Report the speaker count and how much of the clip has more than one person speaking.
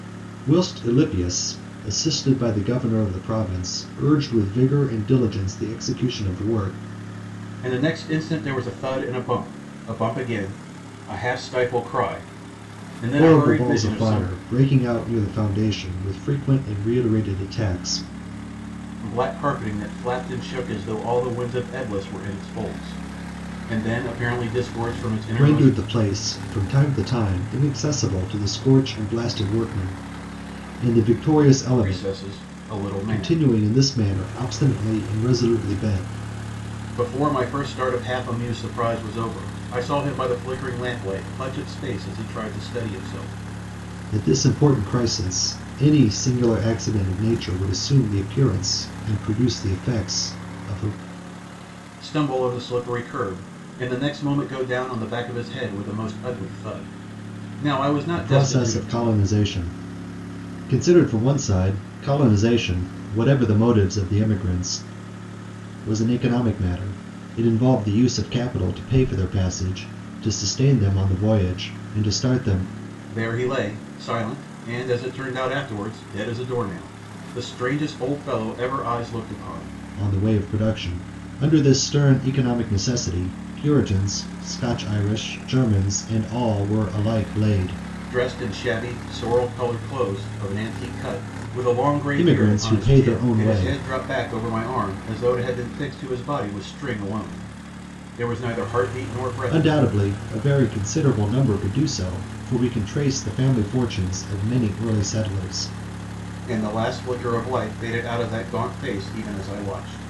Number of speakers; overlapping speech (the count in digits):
2, about 5%